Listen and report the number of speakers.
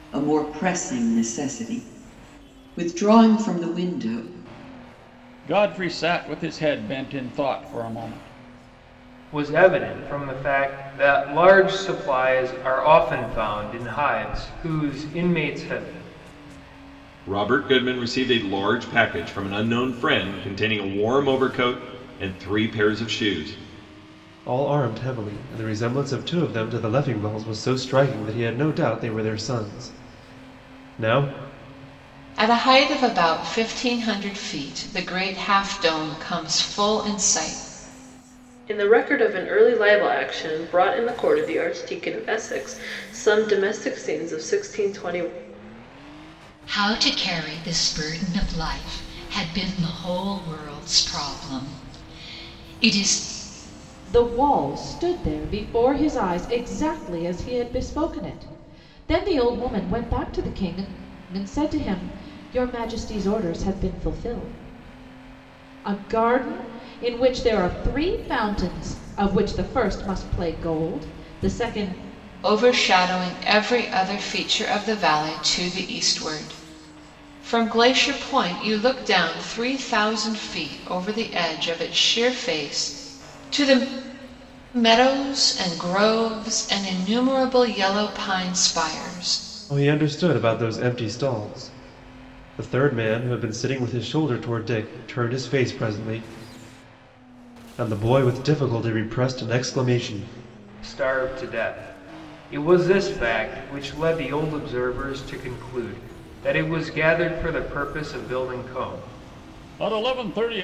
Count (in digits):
9